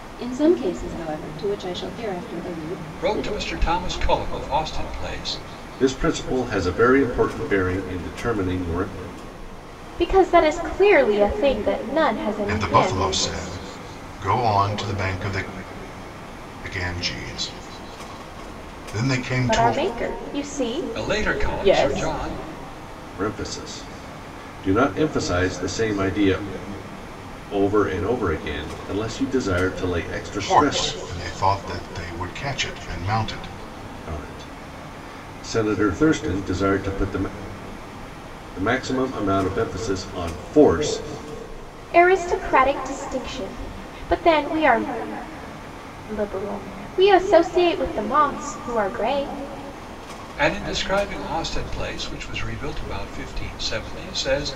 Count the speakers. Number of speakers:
5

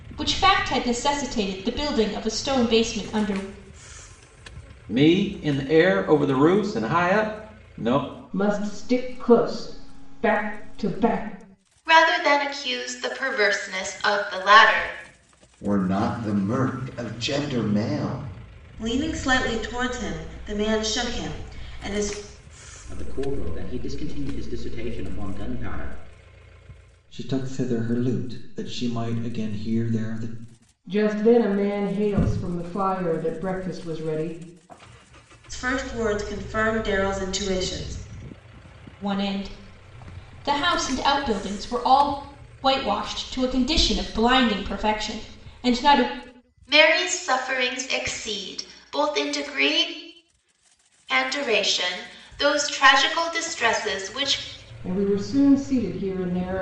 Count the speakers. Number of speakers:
8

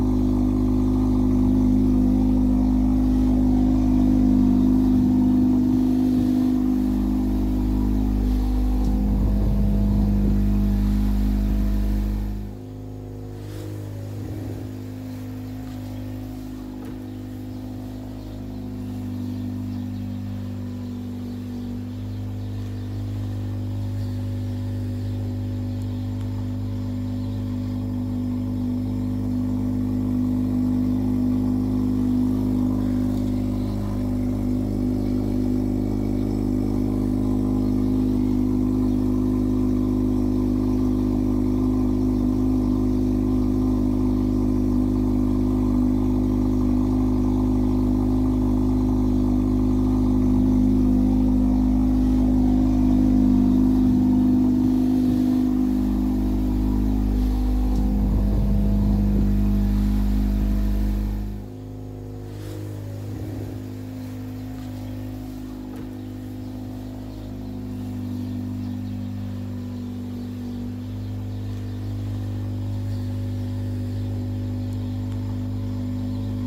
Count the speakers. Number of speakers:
0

